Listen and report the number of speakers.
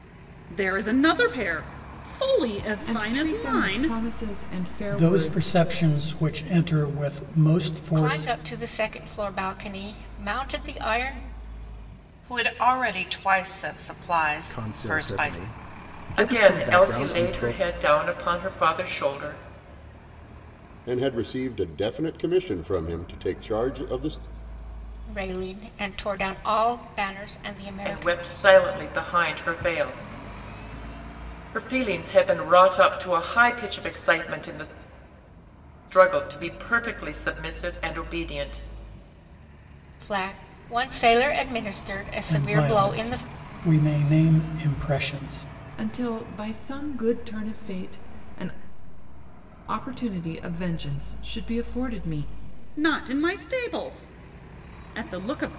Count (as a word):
eight